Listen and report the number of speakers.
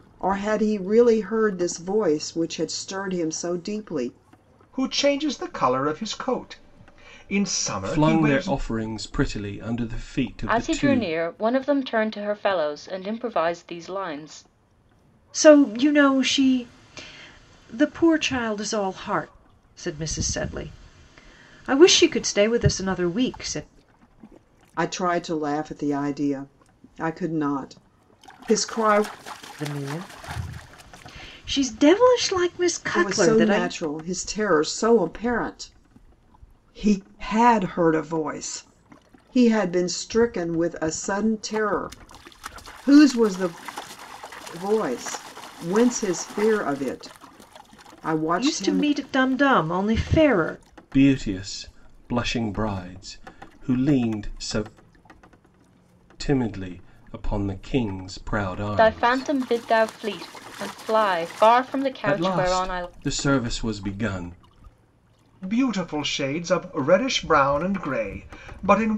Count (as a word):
five